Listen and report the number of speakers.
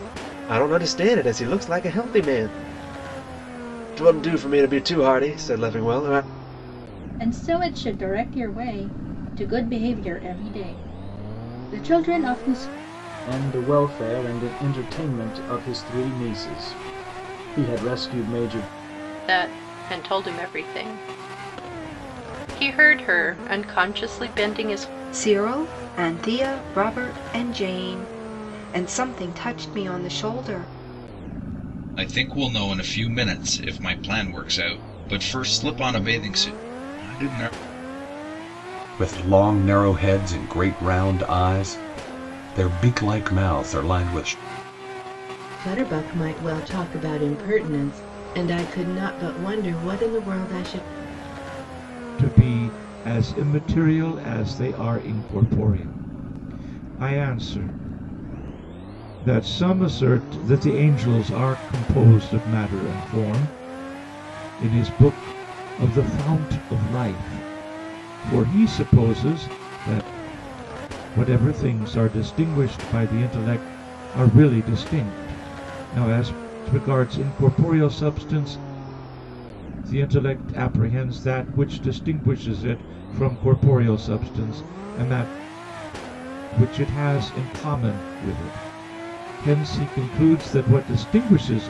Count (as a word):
nine